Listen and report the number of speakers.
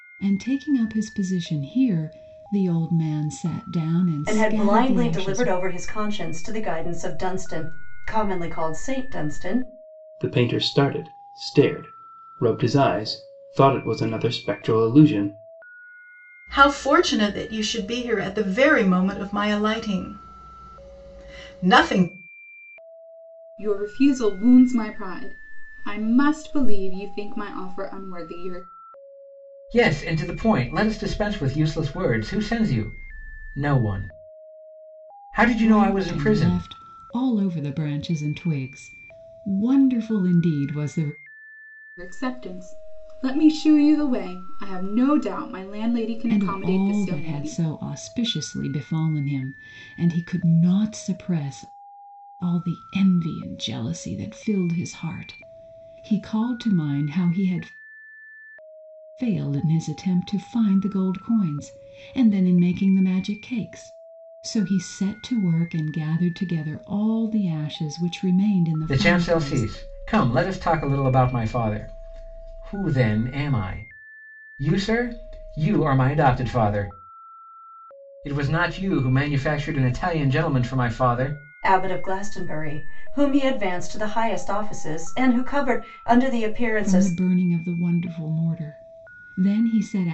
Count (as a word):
six